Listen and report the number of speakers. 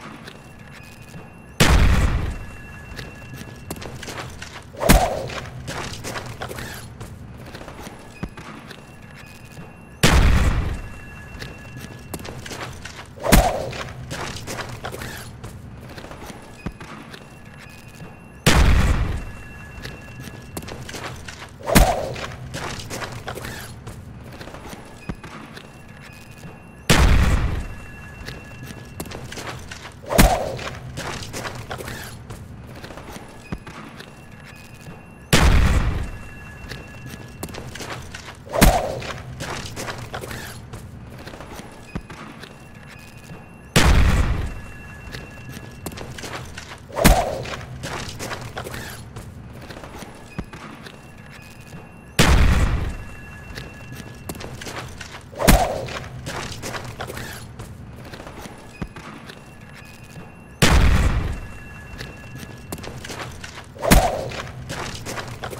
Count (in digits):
0